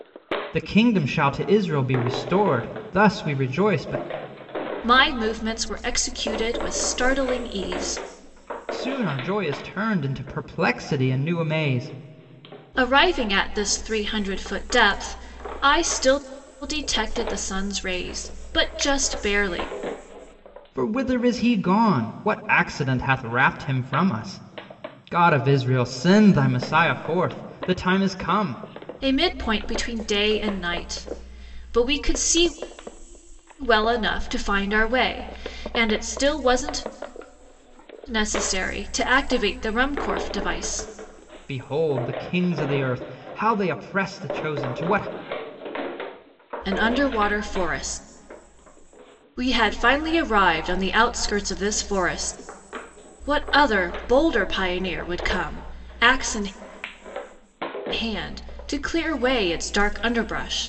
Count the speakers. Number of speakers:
2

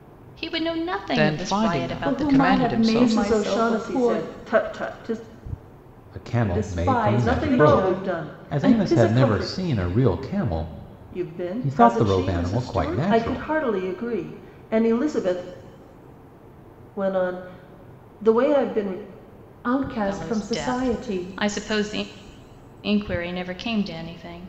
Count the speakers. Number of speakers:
5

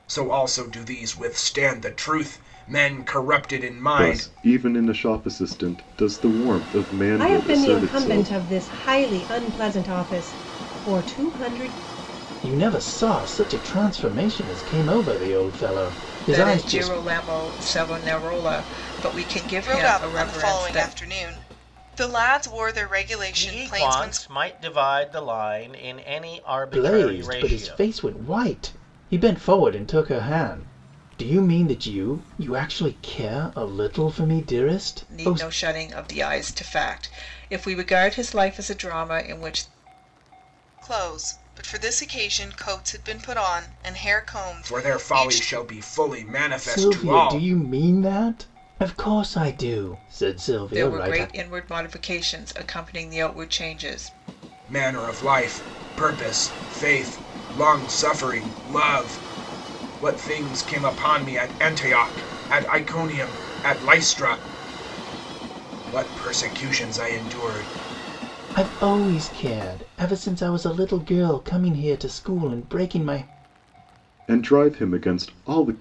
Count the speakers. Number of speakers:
7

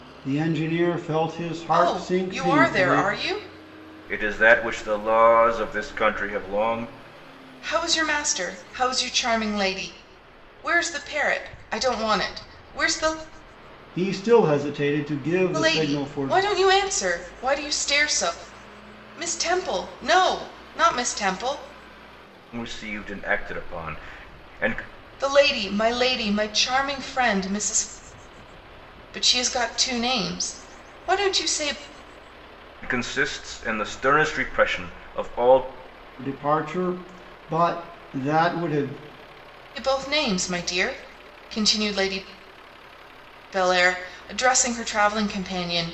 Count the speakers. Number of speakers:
3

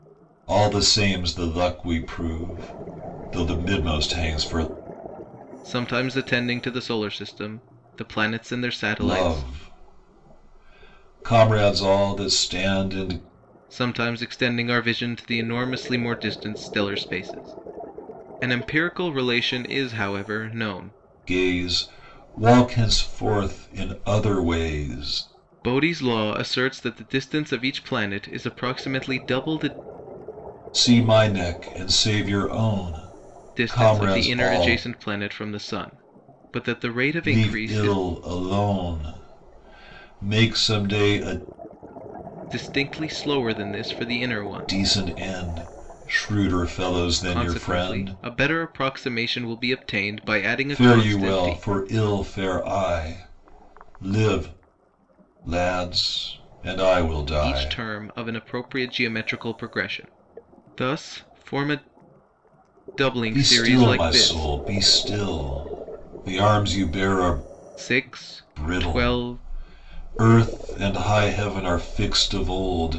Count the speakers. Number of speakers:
2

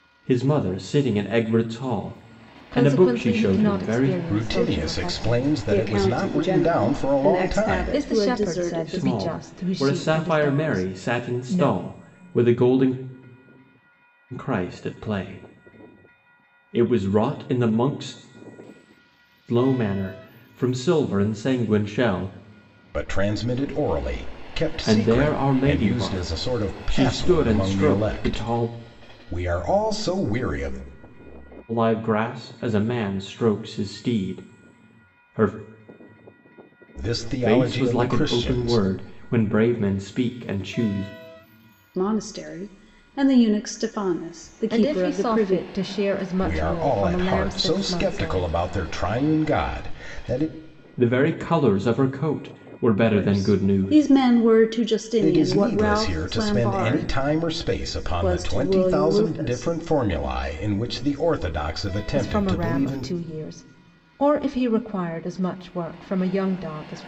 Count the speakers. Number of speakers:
4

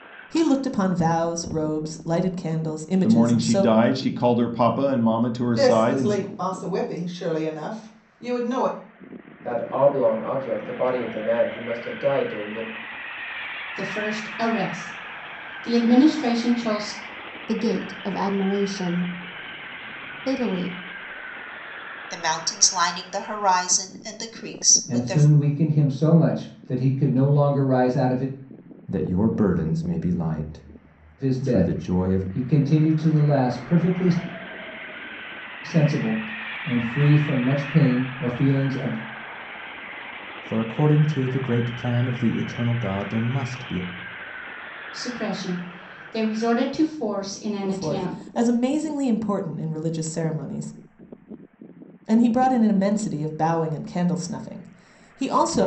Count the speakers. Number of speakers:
9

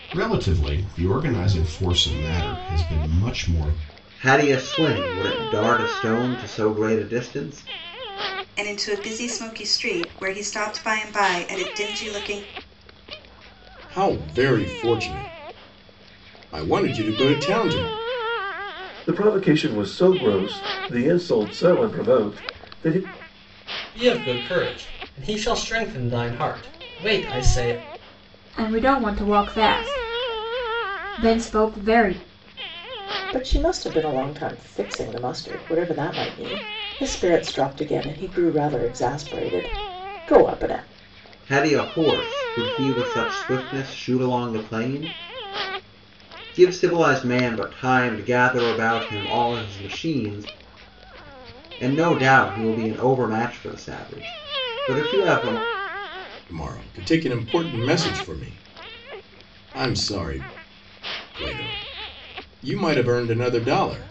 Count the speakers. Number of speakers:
8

